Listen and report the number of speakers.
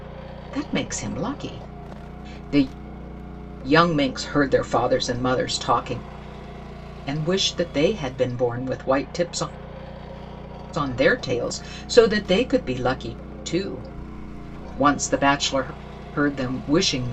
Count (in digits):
1